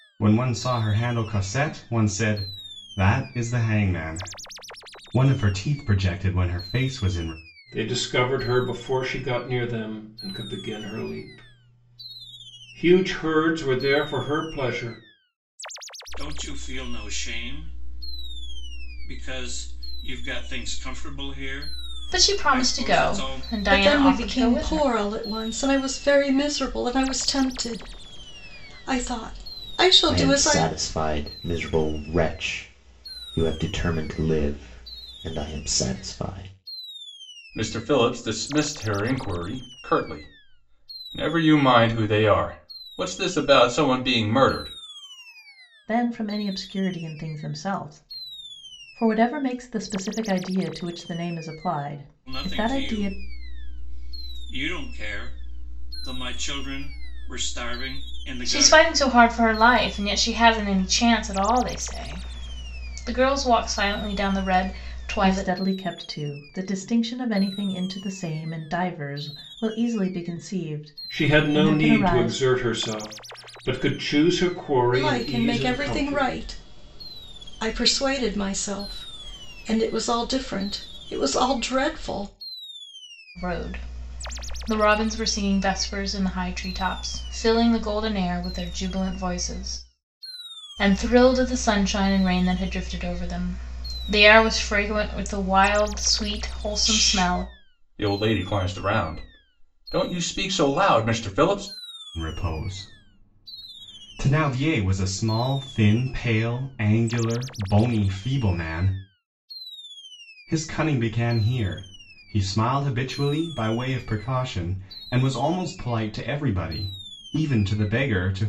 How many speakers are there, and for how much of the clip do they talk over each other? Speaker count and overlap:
8, about 7%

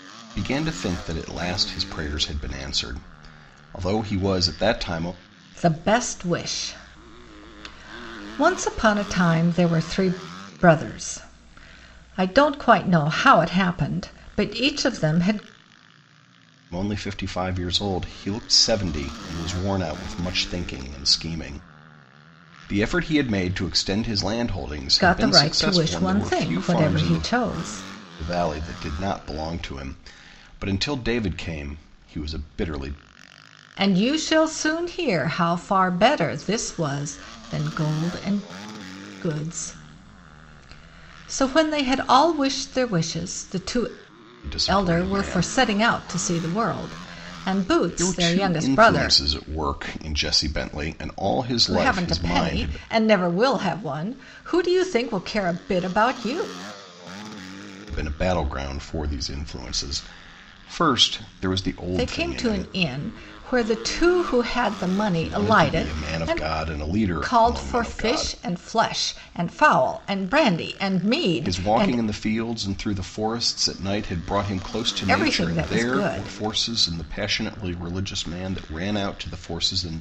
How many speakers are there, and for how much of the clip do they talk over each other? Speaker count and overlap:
2, about 14%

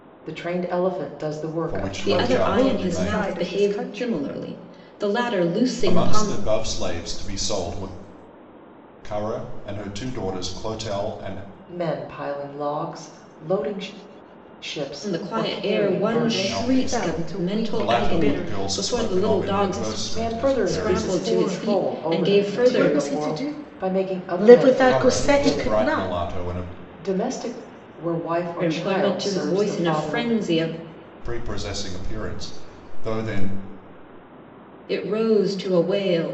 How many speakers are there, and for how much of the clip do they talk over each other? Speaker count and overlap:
4, about 44%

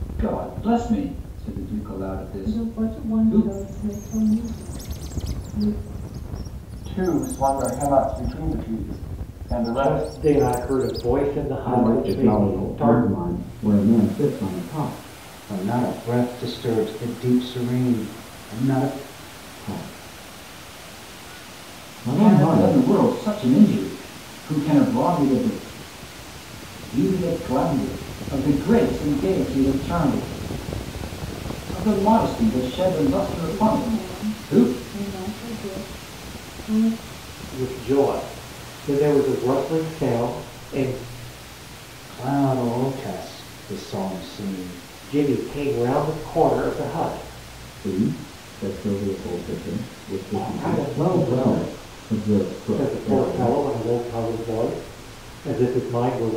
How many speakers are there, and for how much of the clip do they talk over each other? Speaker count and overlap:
6, about 13%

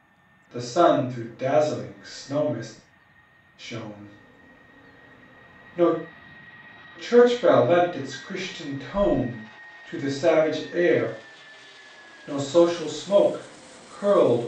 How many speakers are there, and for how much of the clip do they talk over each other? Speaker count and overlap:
1, no overlap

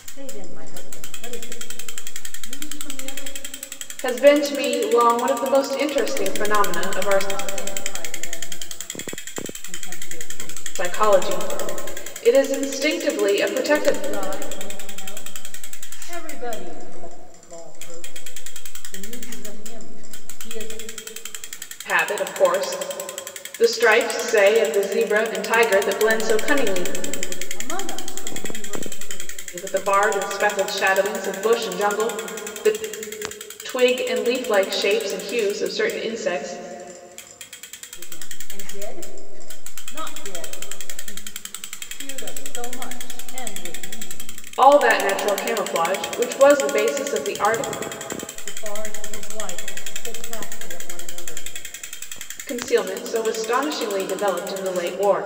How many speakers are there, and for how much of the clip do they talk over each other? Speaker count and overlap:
2, about 7%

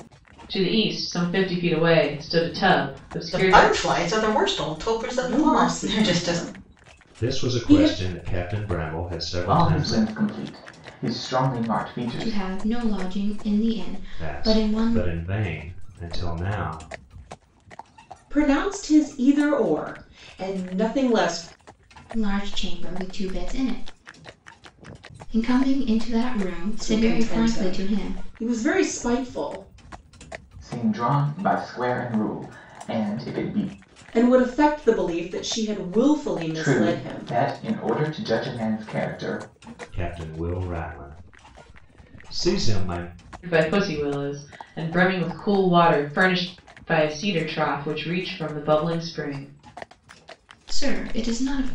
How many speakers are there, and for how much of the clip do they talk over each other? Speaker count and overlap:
6, about 12%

